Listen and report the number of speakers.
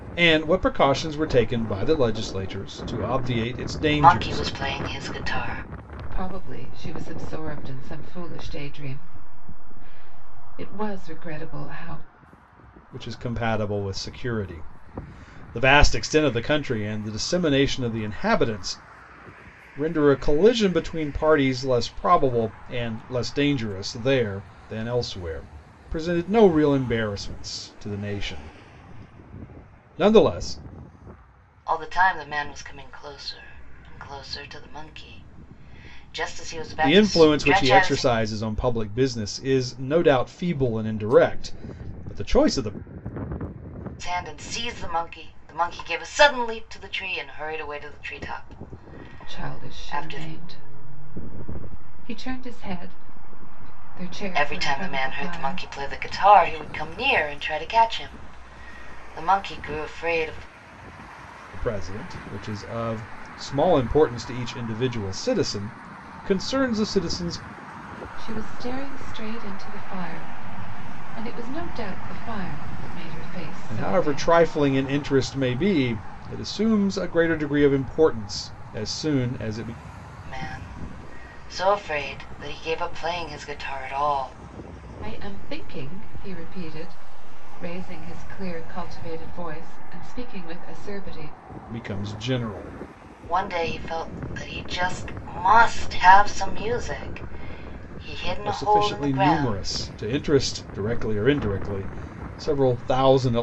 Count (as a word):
three